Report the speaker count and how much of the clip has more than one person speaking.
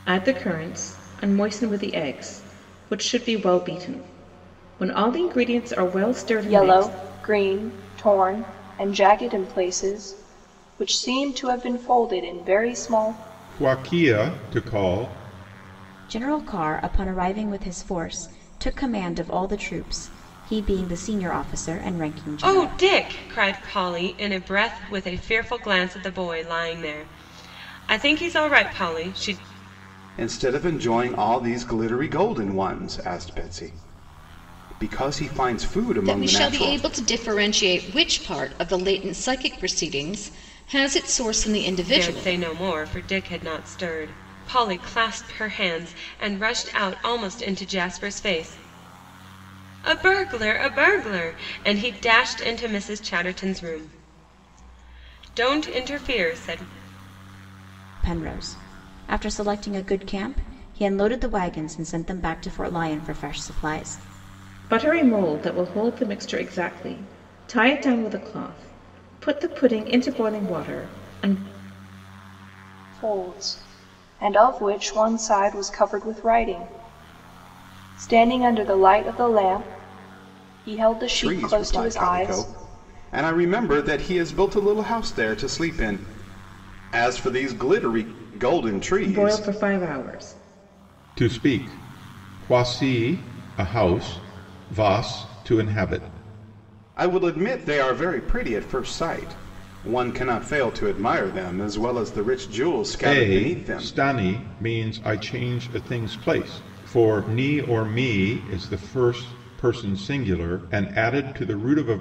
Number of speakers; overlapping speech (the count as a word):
seven, about 4%